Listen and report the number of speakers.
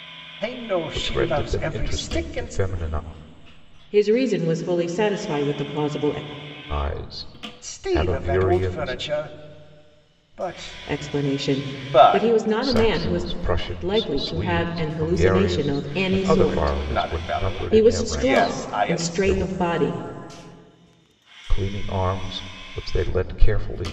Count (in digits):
3